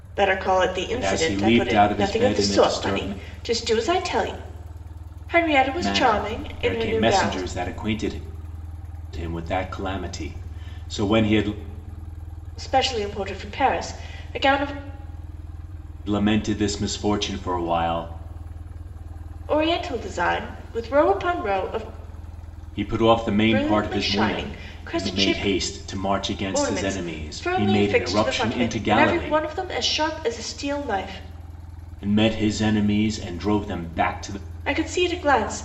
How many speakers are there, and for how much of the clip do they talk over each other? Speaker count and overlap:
2, about 25%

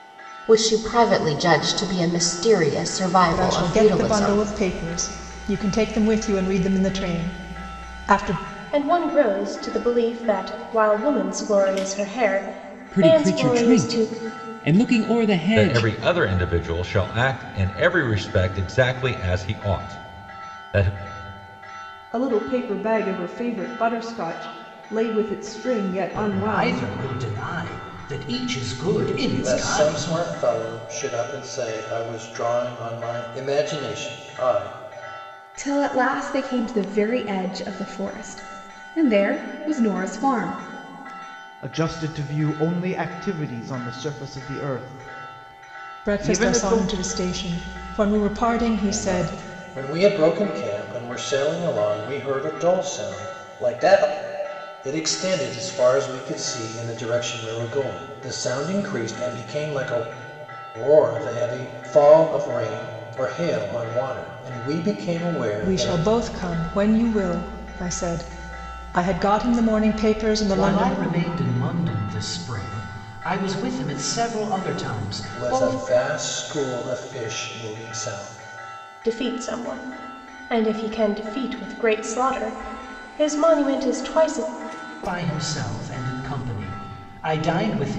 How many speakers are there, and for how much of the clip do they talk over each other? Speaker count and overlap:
10, about 8%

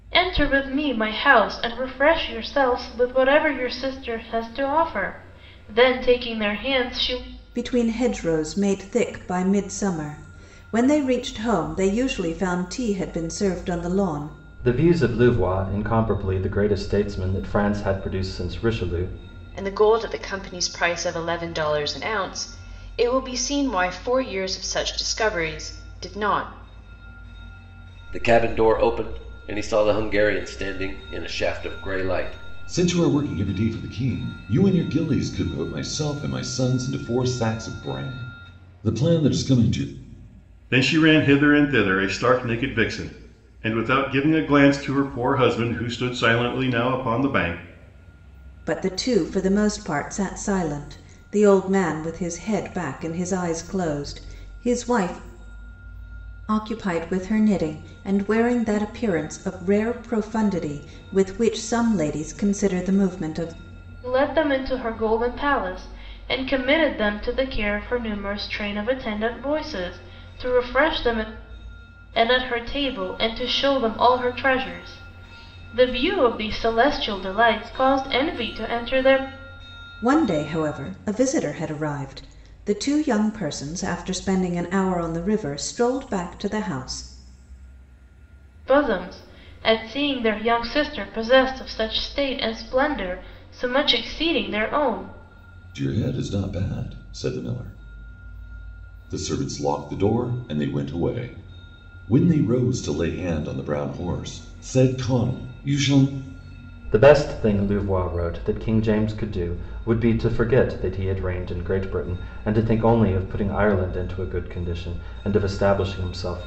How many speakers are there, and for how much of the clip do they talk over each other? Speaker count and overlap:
7, no overlap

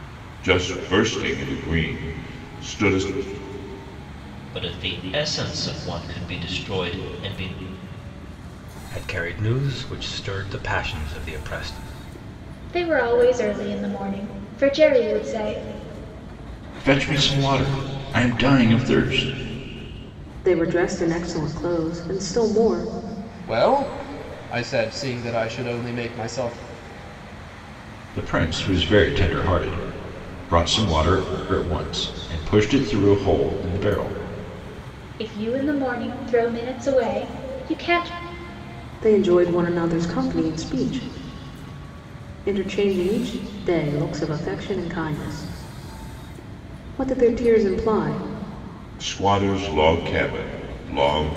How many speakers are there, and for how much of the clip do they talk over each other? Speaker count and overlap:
7, no overlap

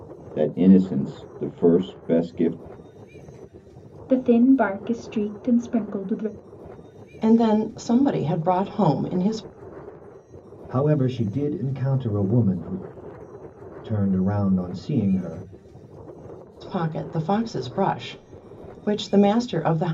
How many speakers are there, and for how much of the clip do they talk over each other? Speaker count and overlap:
4, no overlap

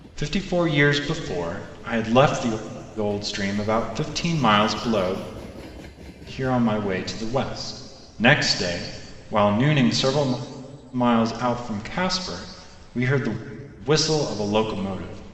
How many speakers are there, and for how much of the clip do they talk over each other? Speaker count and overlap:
1, no overlap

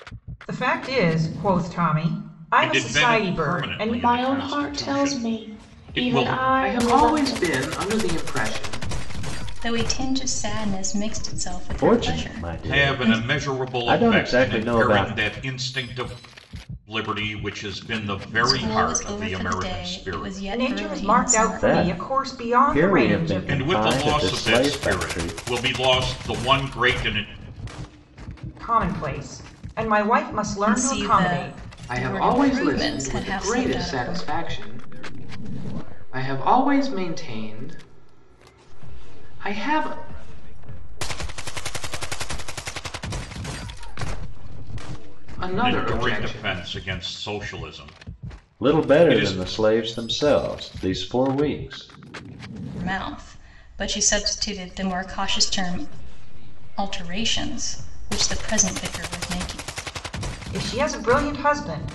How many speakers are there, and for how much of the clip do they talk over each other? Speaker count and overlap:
7, about 48%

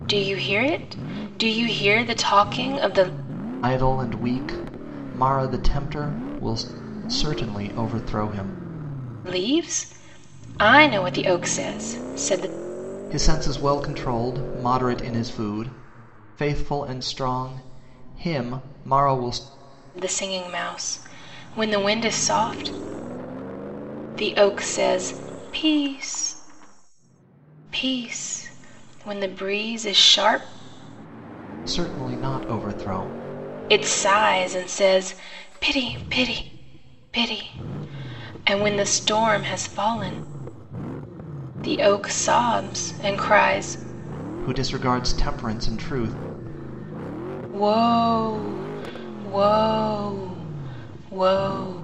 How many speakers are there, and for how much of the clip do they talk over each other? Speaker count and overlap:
2, no overlap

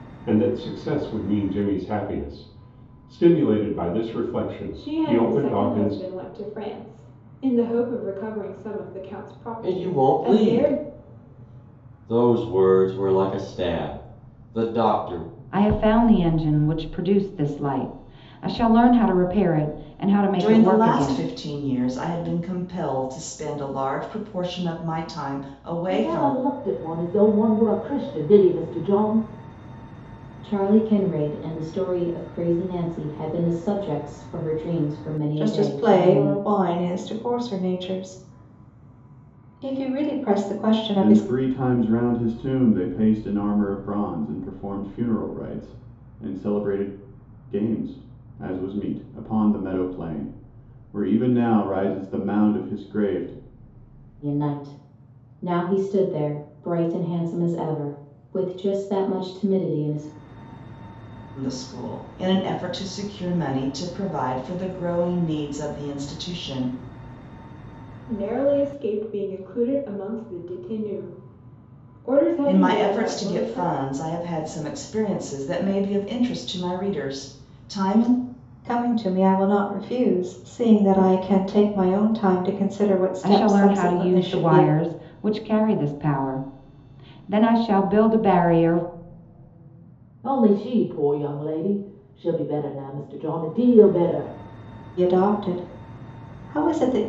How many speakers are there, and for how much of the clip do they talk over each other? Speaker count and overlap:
9, about 9%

